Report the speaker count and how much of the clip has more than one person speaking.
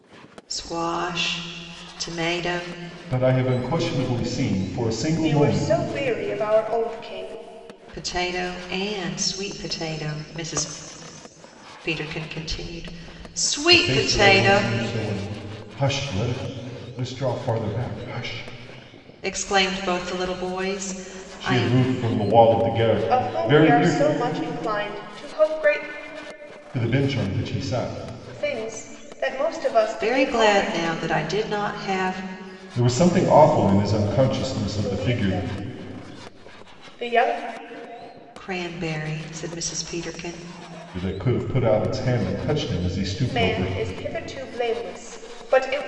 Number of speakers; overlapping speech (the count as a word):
three, about 12%